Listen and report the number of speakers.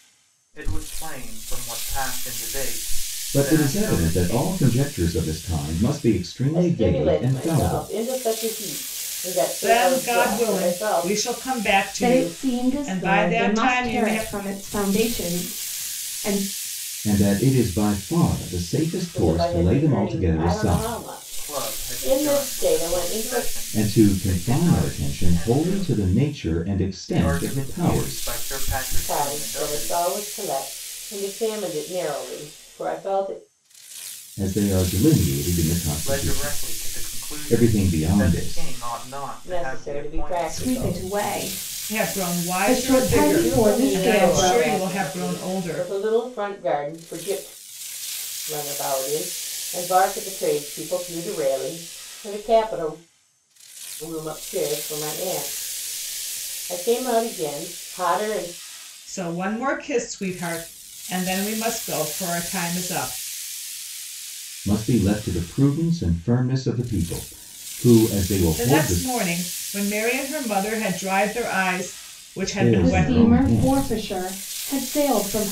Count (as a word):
five